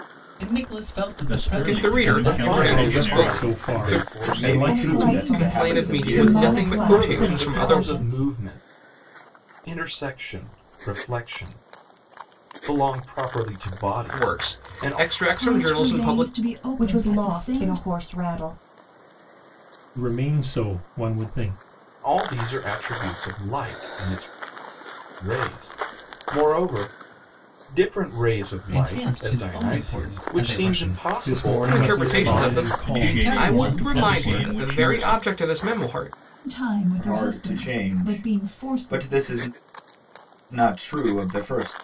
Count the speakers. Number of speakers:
8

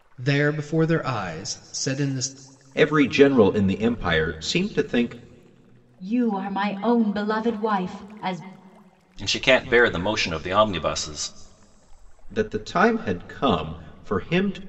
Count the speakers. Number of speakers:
4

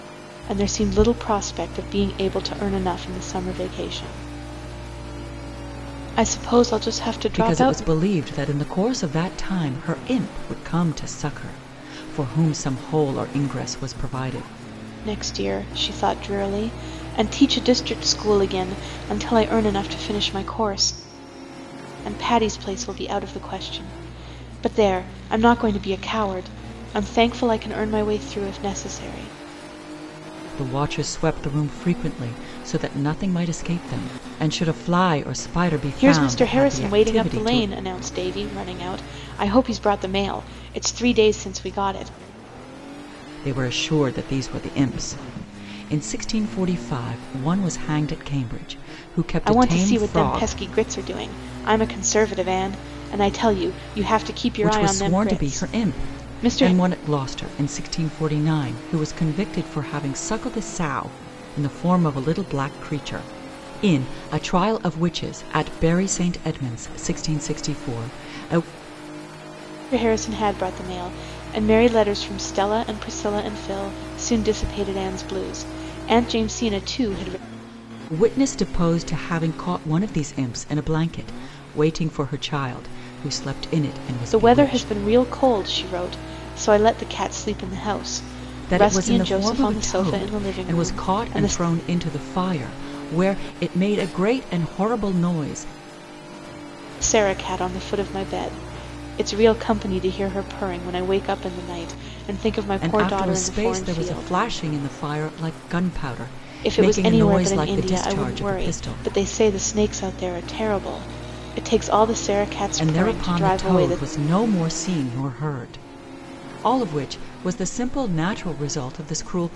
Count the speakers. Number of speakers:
2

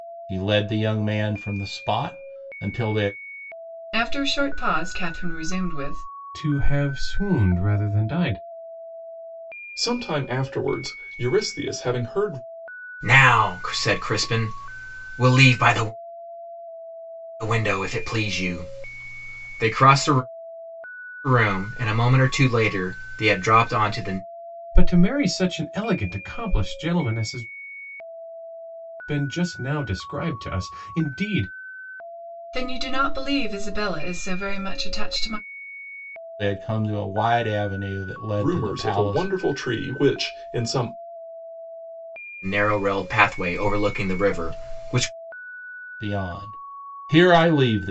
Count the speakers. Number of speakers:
5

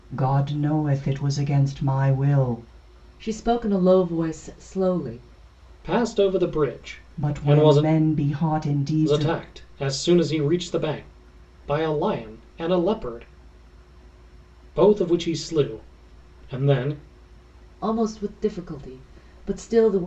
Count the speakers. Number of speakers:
3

